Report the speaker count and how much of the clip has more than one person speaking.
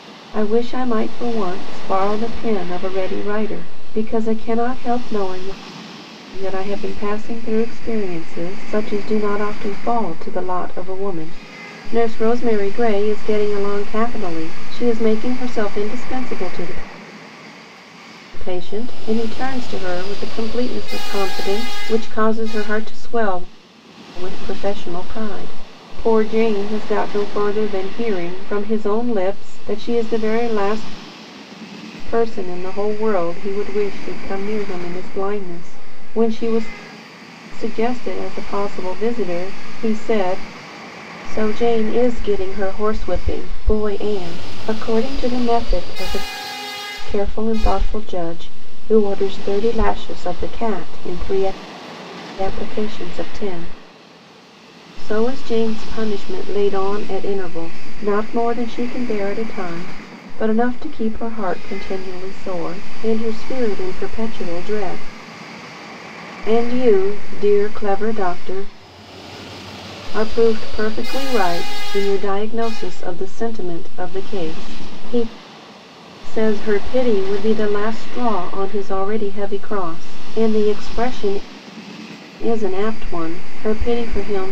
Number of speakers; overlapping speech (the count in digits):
1, no overlap